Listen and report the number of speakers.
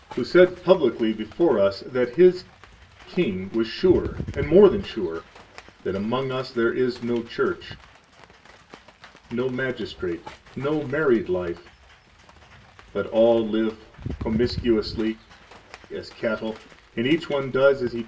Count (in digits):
1